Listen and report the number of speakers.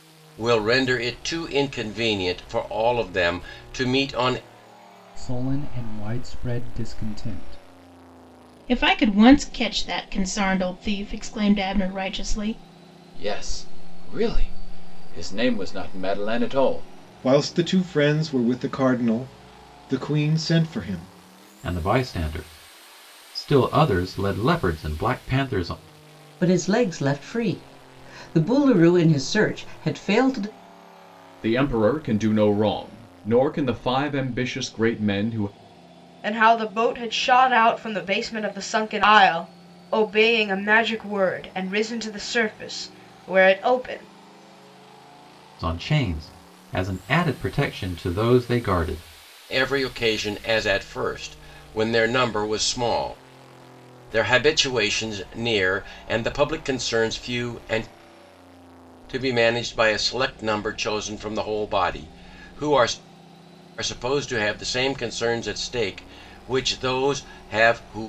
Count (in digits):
9